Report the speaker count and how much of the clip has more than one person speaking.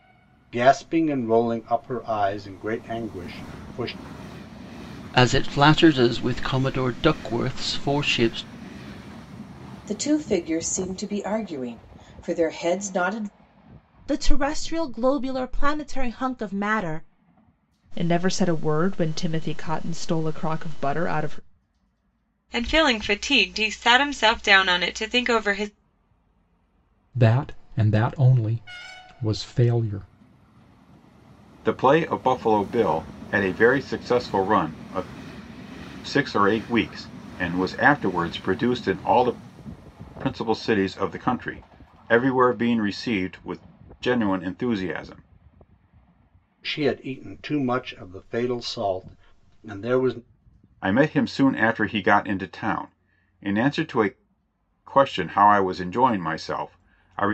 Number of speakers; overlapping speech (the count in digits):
8, no overlap